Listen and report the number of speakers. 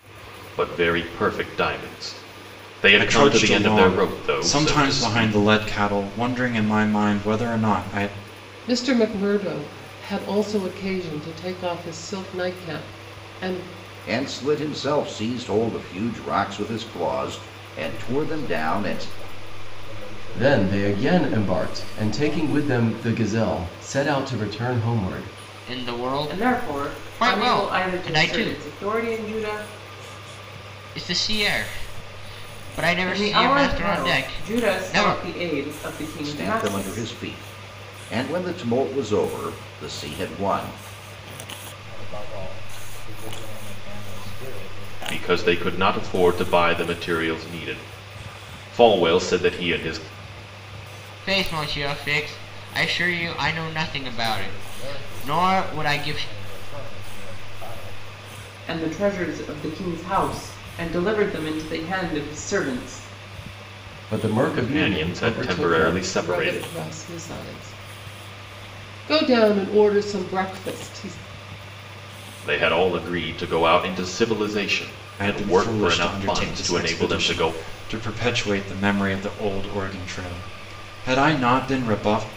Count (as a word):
eight